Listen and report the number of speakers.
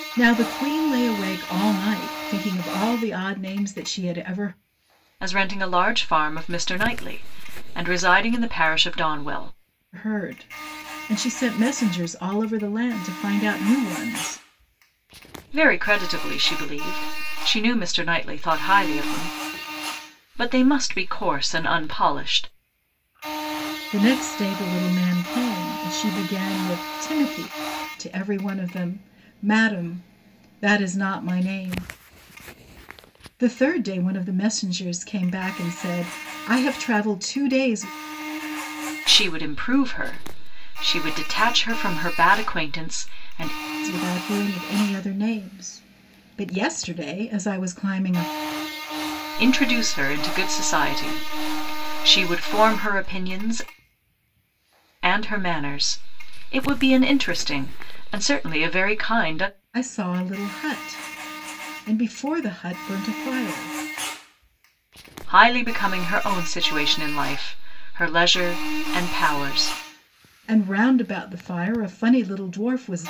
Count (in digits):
2